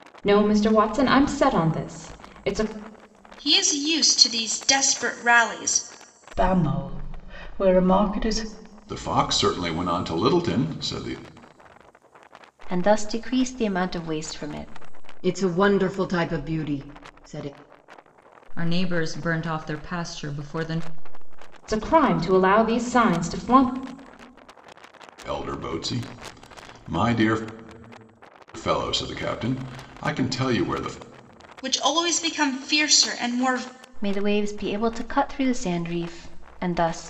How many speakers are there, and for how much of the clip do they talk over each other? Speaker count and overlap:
7, no overlap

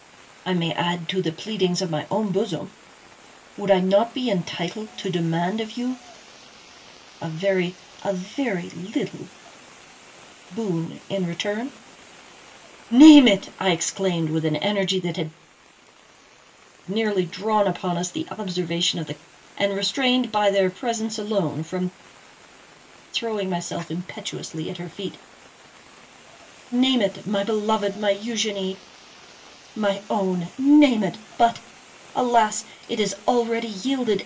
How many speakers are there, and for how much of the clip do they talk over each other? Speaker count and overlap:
1, no overlap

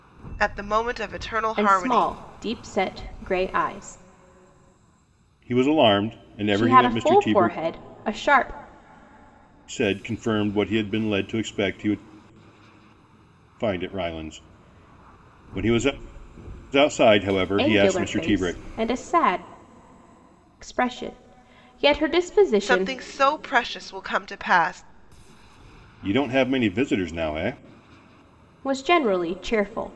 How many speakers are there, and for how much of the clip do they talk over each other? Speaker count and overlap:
3, about 11%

